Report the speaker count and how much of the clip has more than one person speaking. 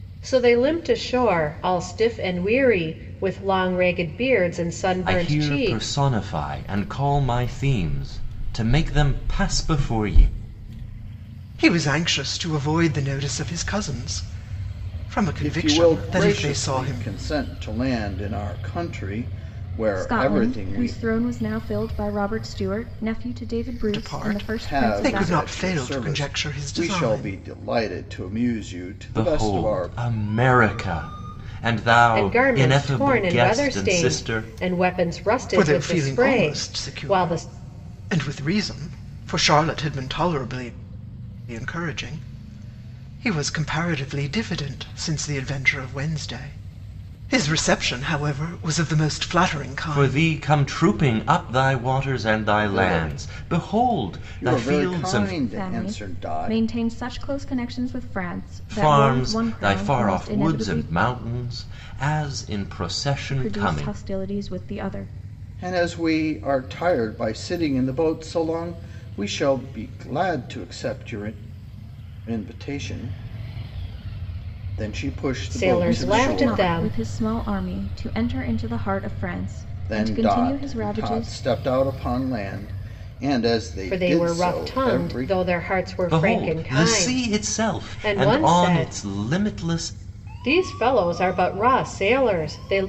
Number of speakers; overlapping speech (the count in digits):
5, about 29%